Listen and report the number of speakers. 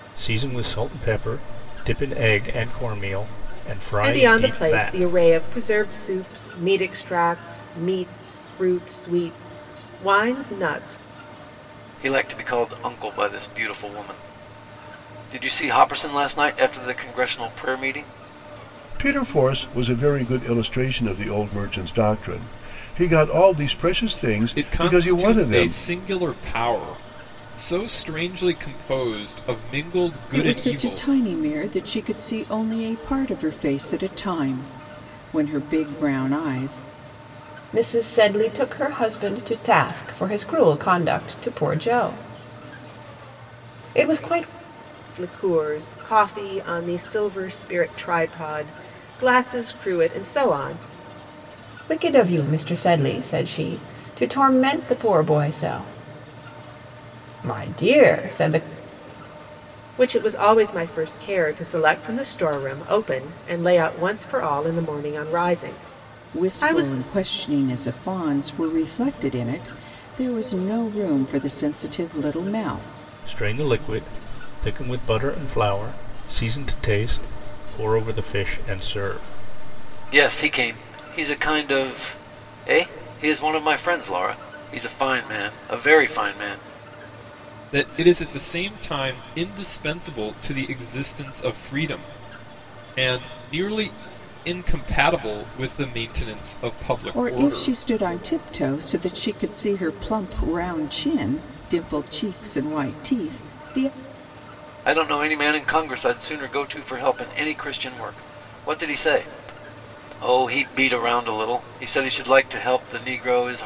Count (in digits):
7